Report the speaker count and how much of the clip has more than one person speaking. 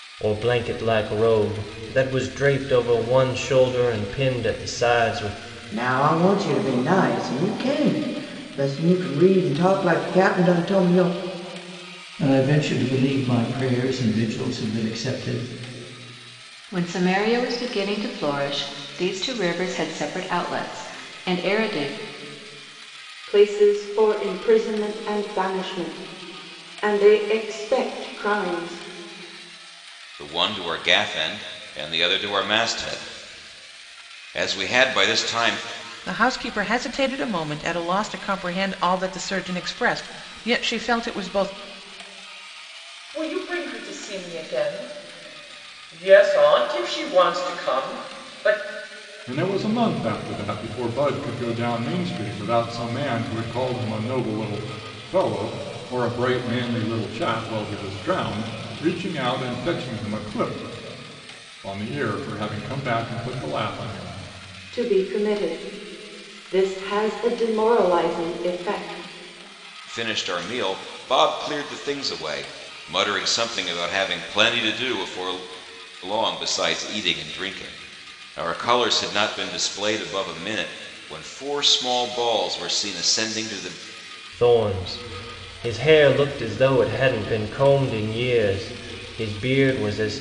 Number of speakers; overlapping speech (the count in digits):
9, no overlap